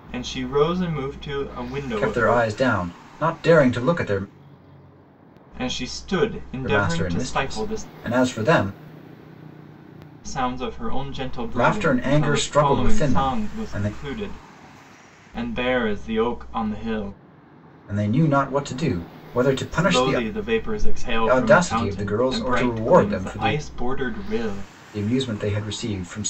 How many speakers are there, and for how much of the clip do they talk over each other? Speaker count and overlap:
two, about 26%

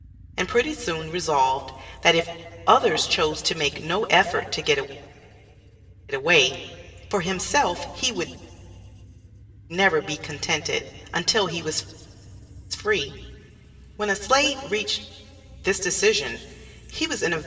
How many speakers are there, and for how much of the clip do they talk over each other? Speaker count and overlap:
one, no overlap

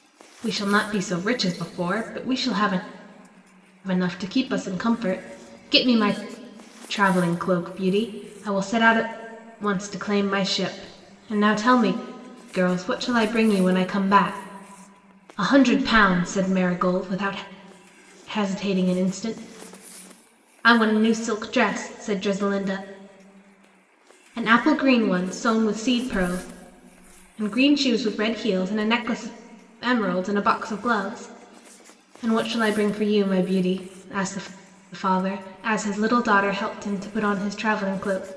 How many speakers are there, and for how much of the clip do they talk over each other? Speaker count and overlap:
one, no overlap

